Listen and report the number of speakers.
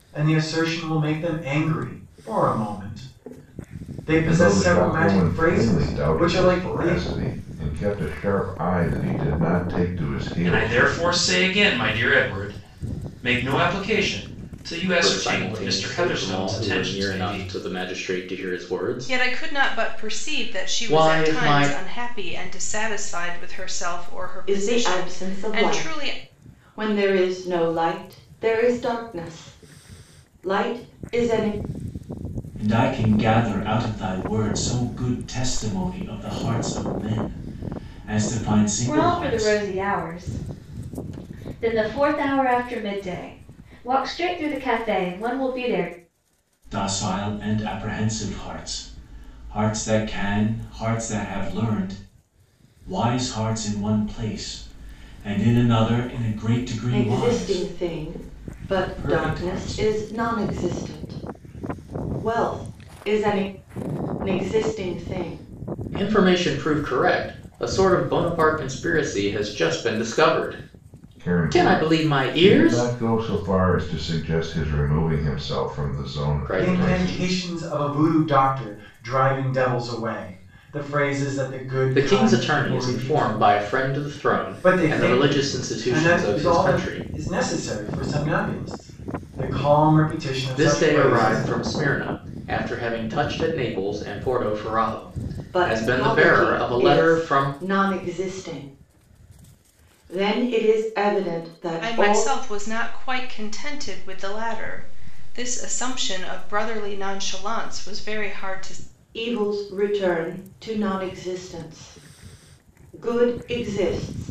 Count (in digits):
8